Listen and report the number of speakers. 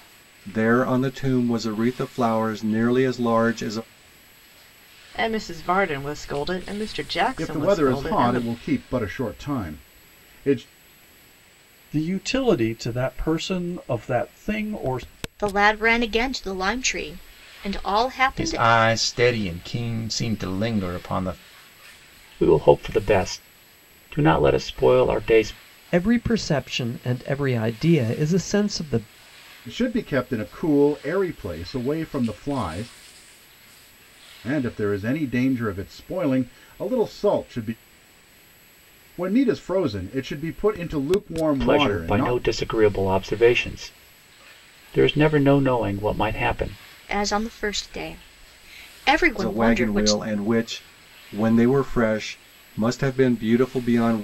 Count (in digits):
8